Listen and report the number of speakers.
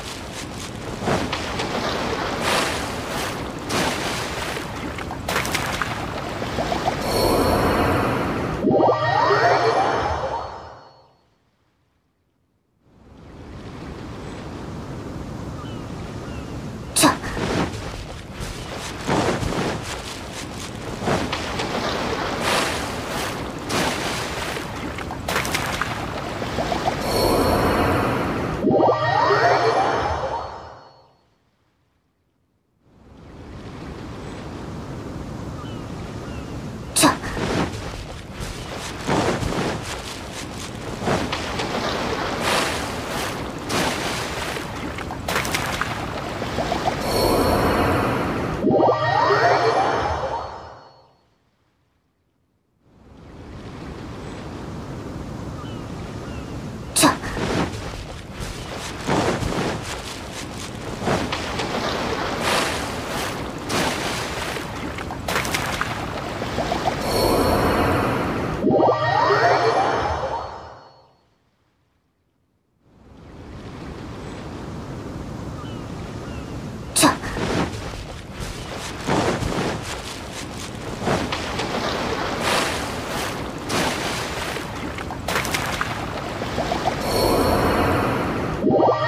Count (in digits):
0